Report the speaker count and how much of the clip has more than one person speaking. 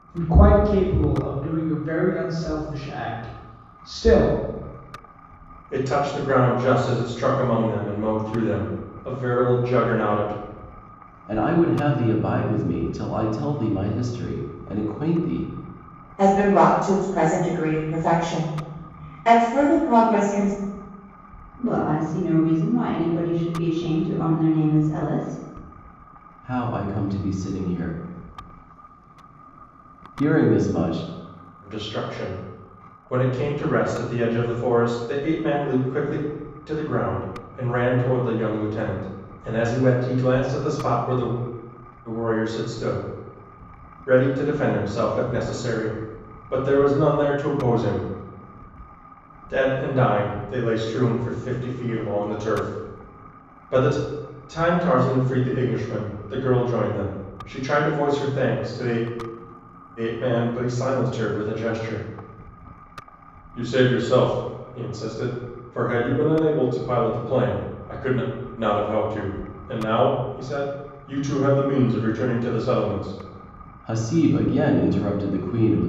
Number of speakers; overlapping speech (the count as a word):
five, no overlap